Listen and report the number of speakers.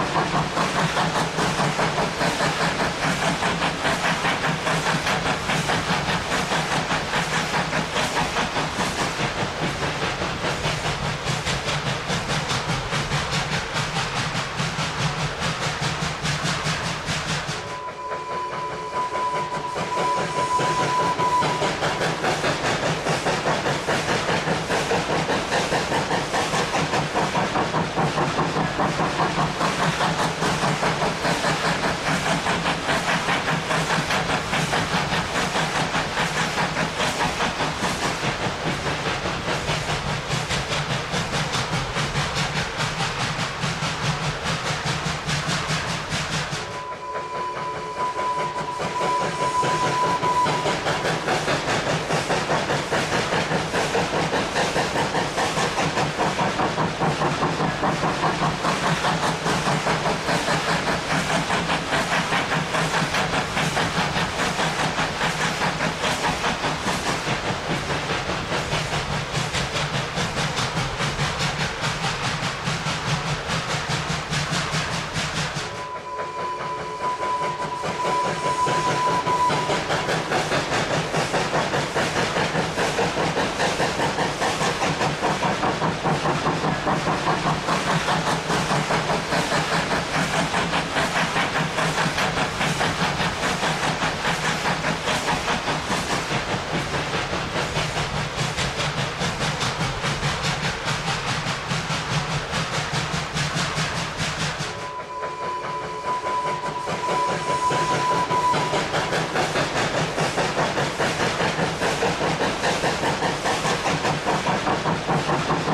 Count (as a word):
zero